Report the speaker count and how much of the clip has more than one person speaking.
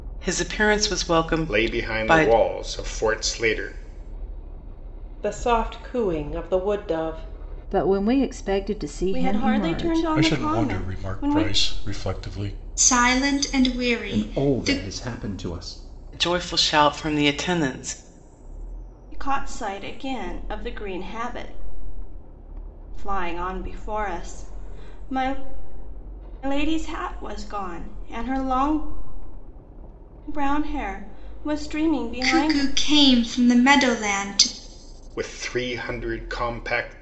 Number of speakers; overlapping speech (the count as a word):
eight, about 12%